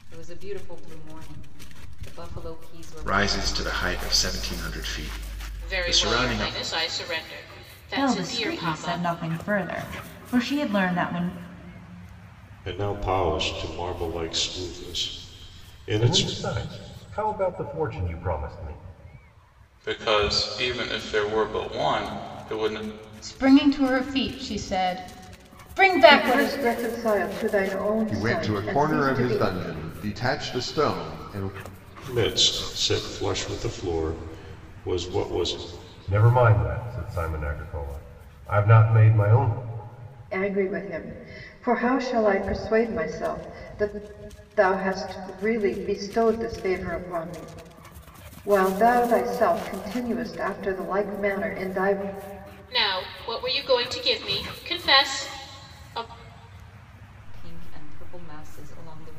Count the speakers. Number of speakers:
10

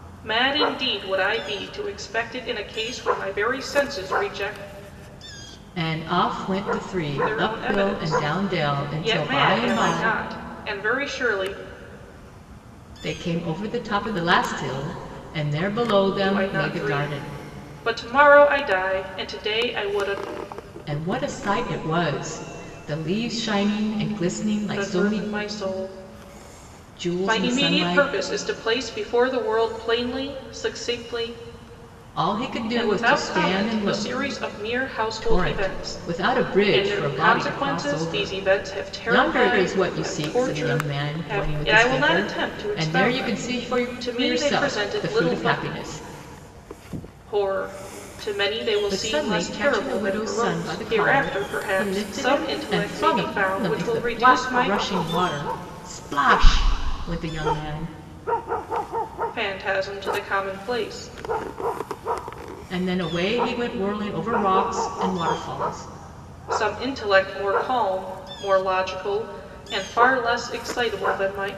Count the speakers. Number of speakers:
2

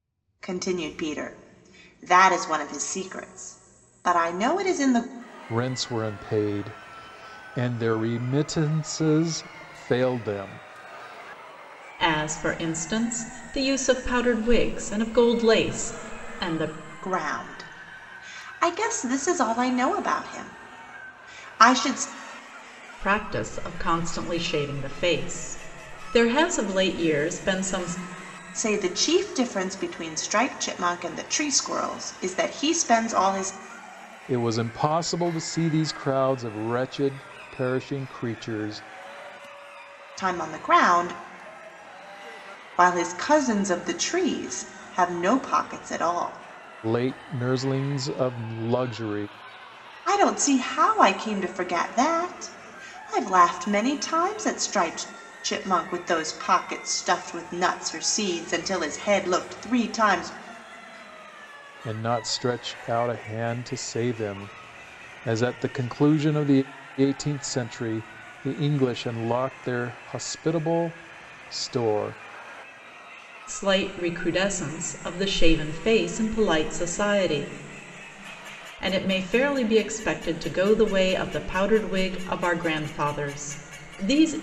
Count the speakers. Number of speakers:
3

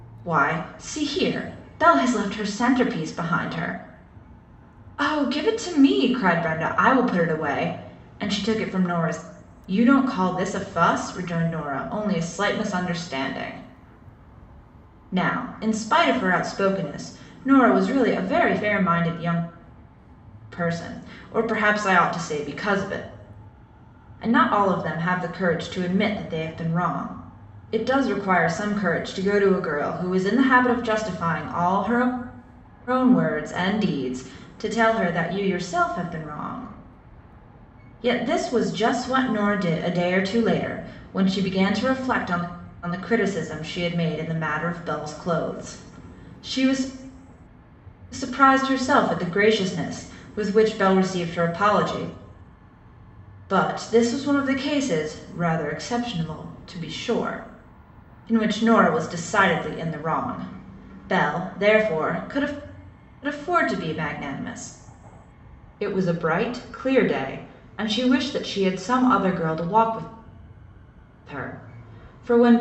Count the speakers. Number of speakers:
1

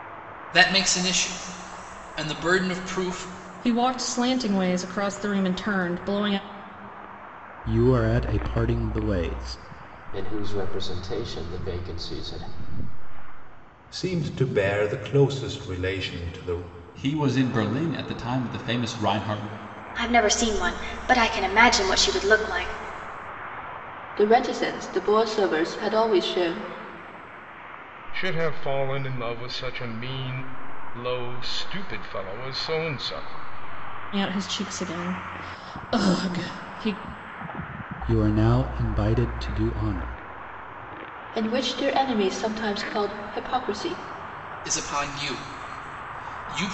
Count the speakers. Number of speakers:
9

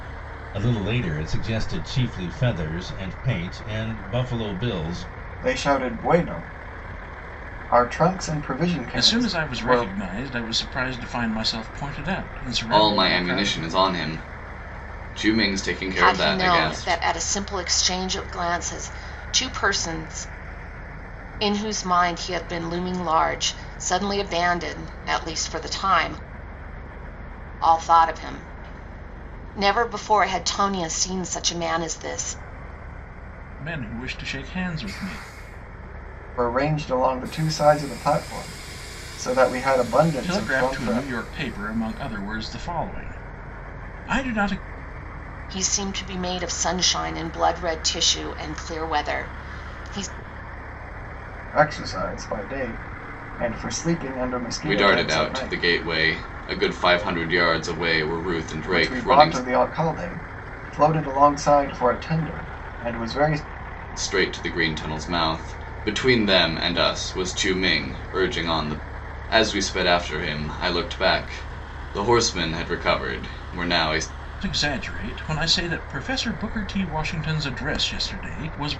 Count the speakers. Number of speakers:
5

